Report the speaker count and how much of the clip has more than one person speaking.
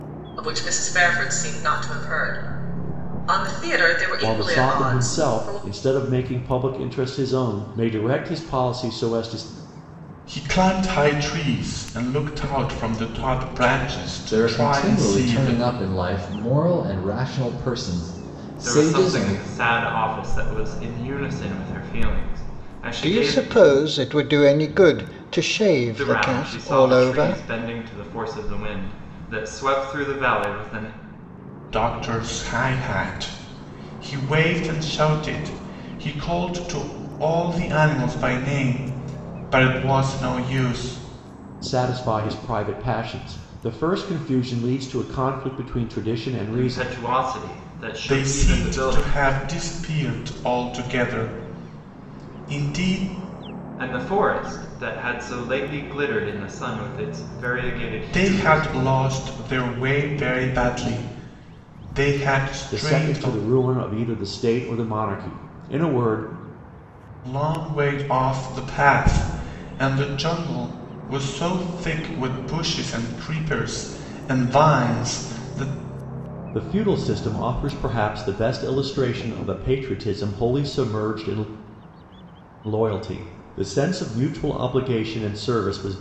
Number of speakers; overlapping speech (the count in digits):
6, about 10%